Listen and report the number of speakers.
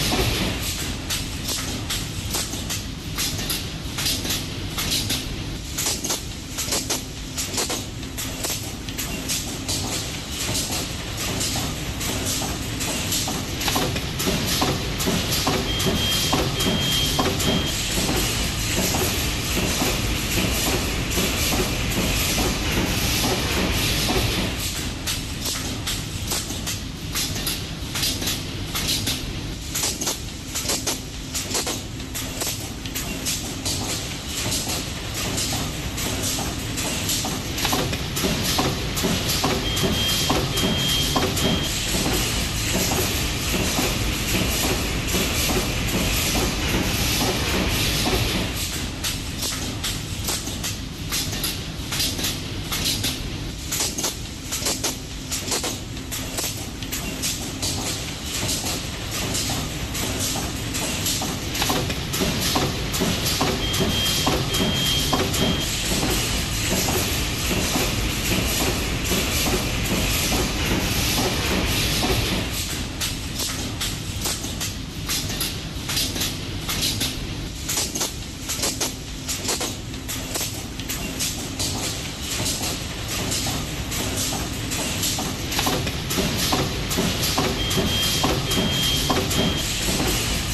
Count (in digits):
0